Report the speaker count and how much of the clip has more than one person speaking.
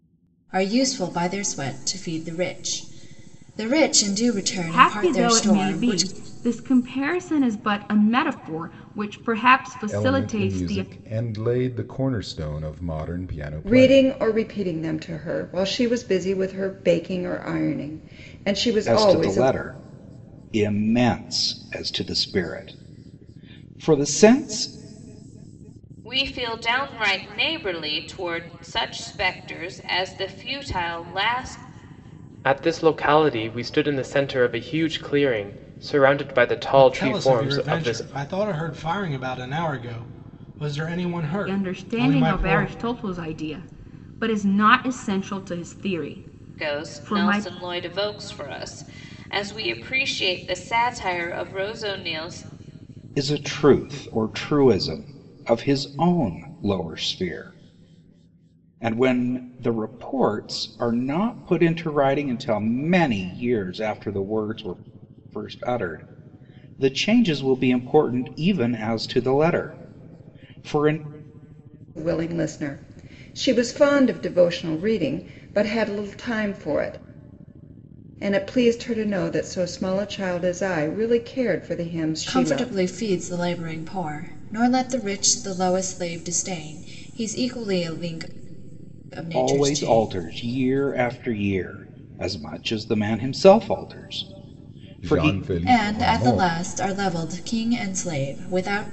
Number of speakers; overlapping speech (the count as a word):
eight, about 10%